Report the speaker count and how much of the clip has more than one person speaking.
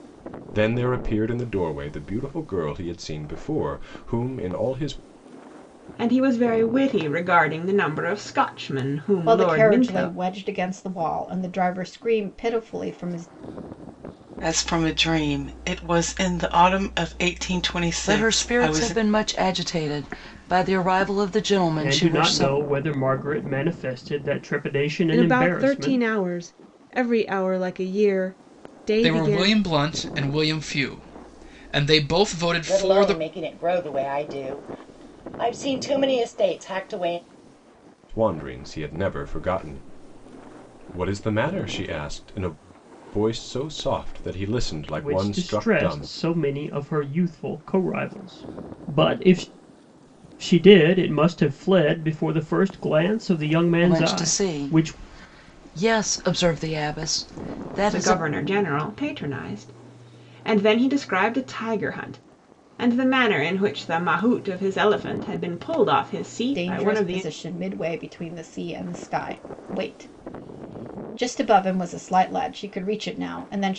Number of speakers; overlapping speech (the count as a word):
nine, about 11%